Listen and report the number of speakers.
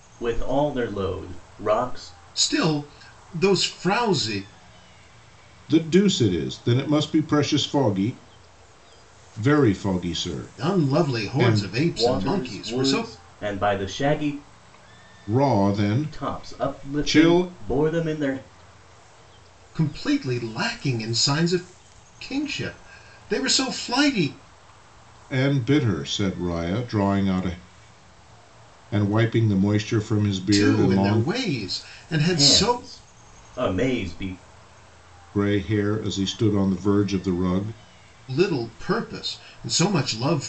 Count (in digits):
3